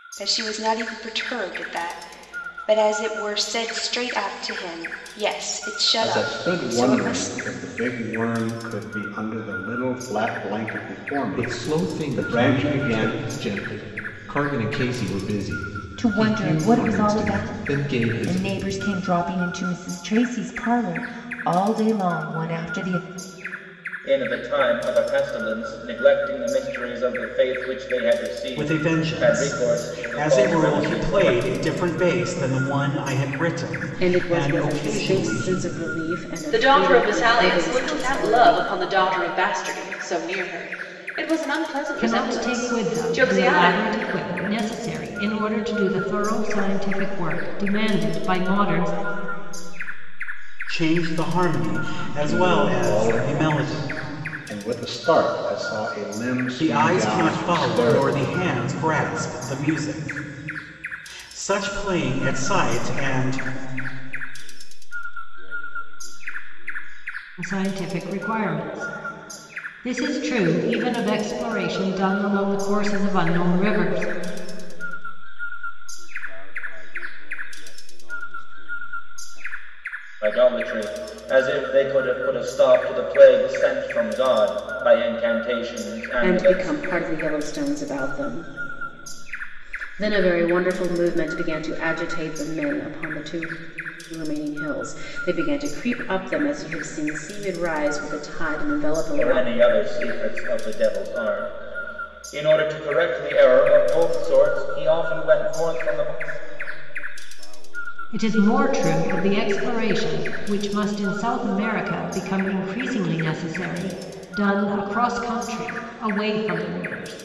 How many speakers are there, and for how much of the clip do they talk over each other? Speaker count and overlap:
10, about 29%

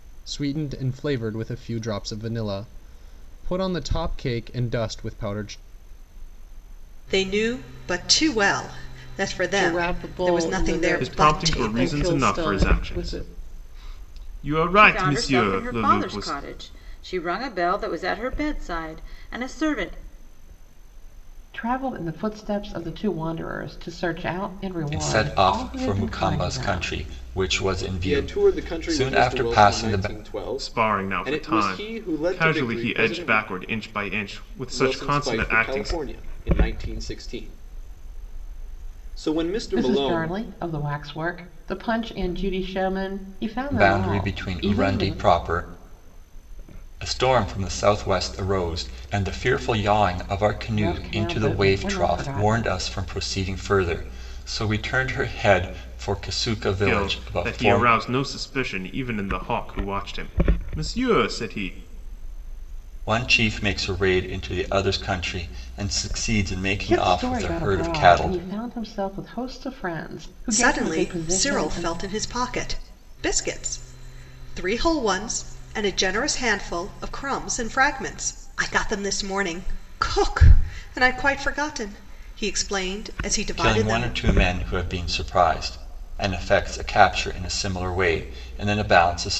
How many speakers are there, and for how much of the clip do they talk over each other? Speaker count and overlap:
8, about 25%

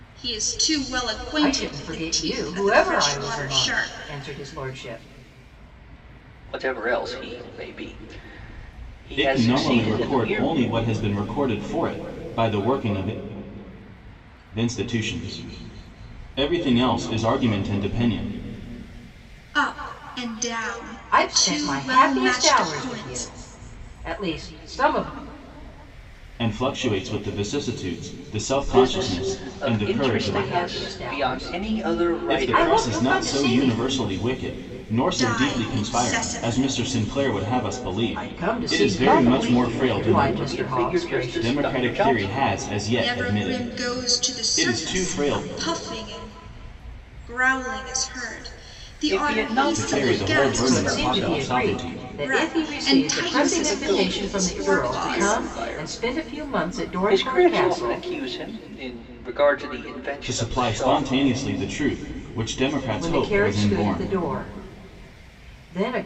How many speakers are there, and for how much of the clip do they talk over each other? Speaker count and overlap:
4, about 45%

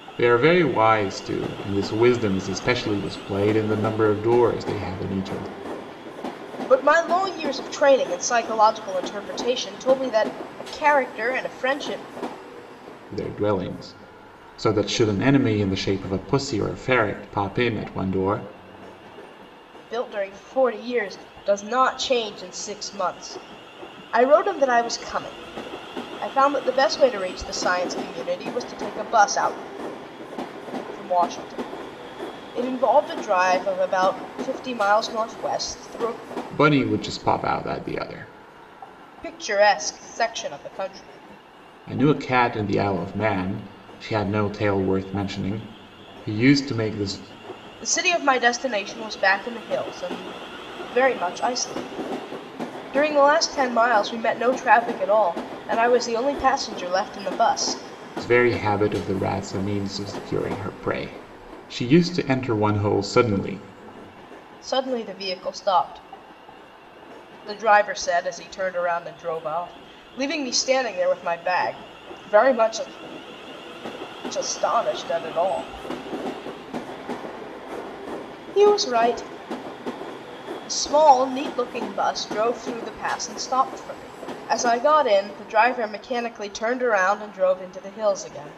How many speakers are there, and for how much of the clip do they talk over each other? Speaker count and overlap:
2, no overlap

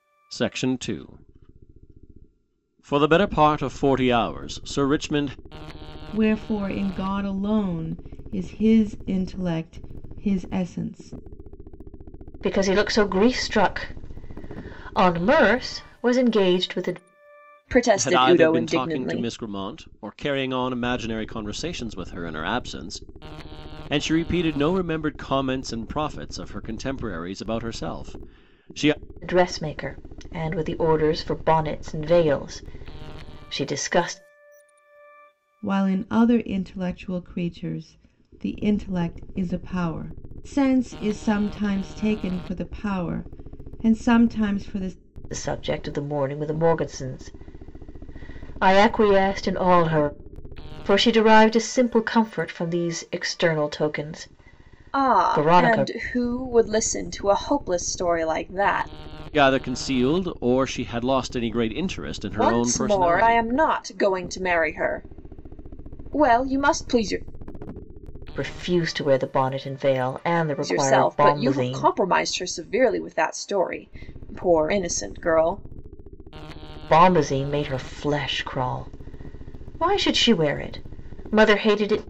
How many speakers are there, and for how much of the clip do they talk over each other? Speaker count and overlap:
4, about 6%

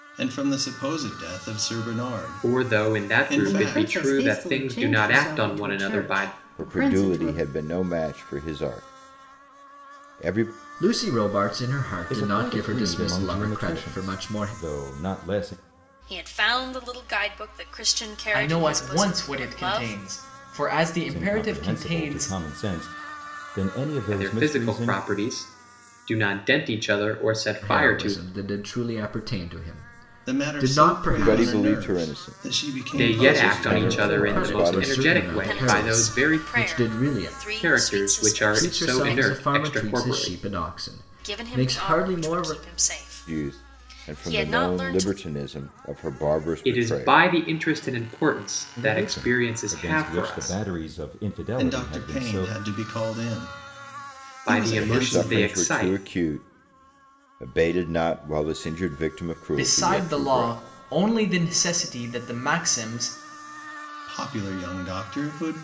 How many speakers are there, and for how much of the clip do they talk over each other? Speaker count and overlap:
8, about 48%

